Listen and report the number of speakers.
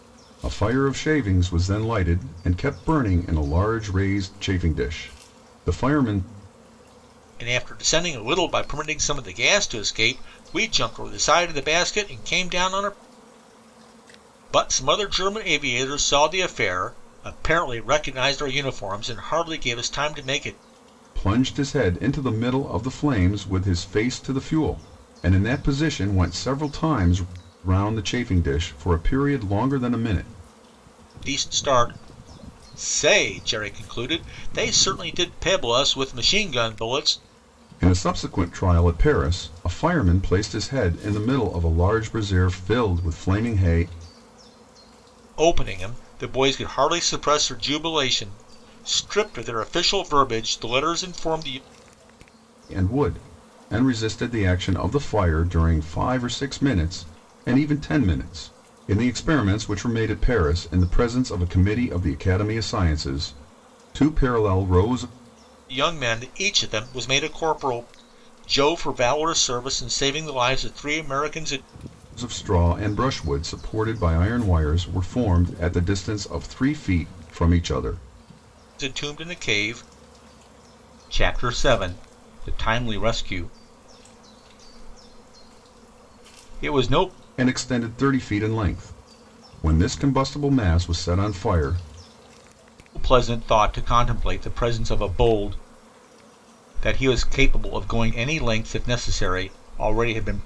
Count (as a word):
two